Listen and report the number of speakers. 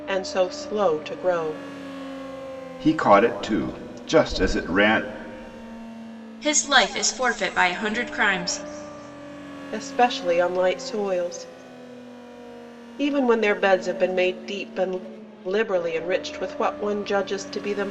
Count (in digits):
3